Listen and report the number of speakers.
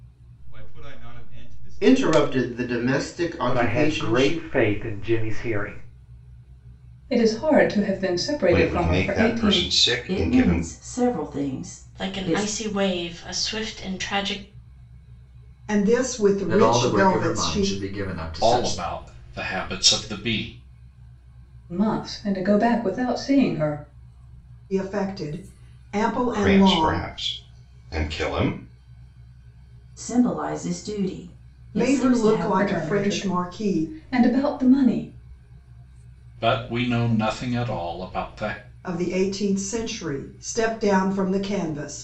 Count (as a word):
ten